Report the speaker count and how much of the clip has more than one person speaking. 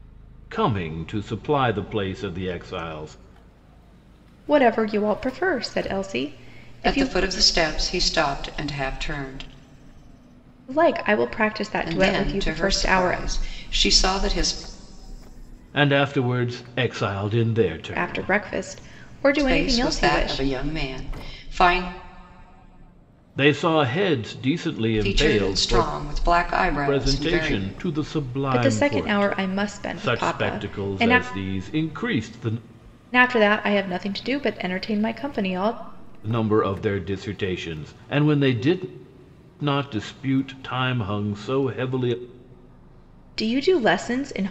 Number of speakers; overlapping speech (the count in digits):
3, about 16%